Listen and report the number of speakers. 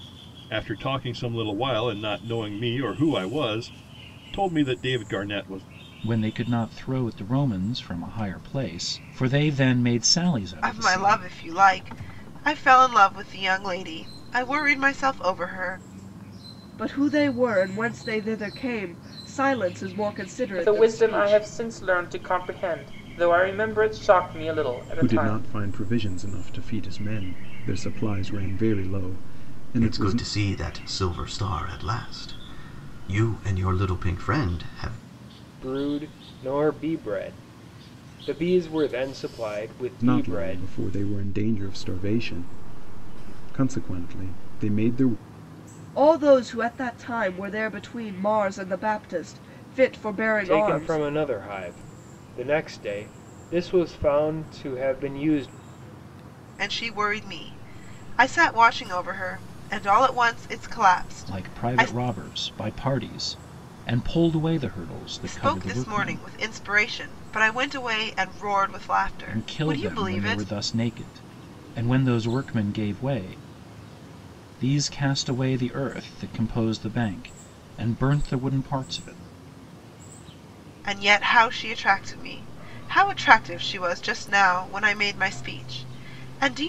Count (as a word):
eight